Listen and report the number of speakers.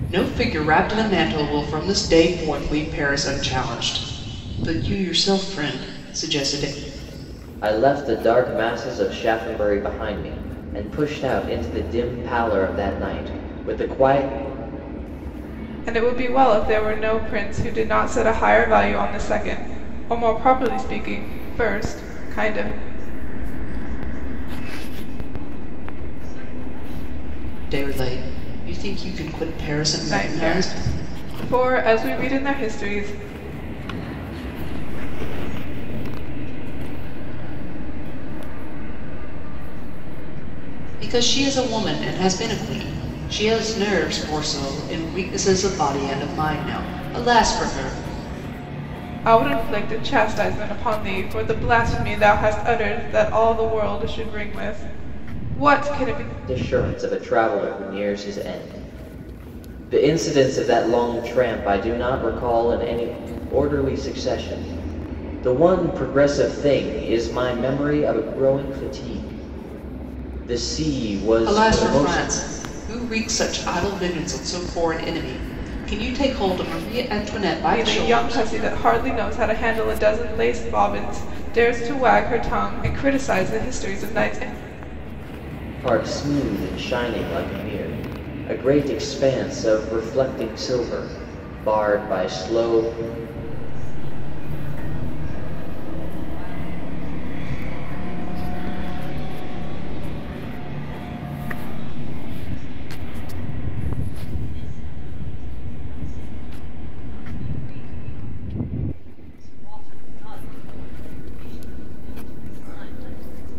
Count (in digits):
4